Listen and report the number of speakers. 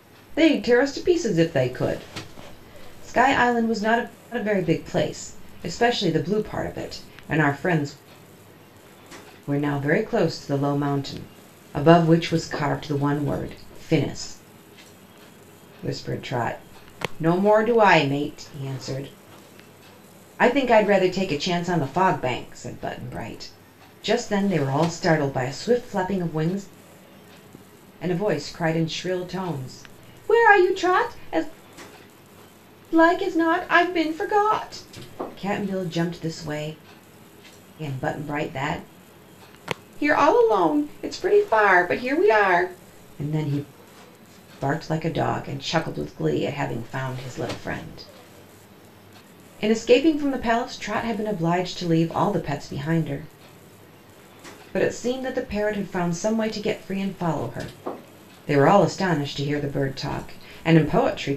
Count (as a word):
one